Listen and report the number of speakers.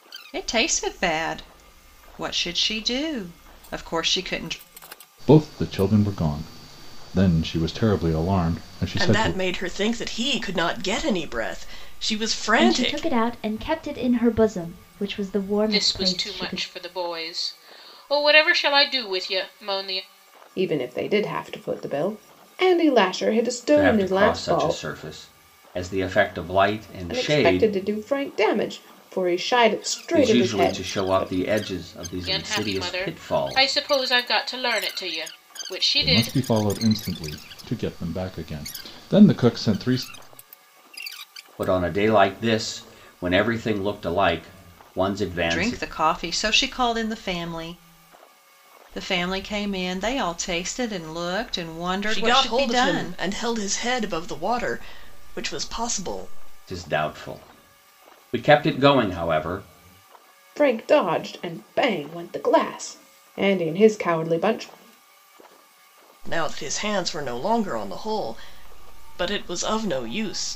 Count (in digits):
7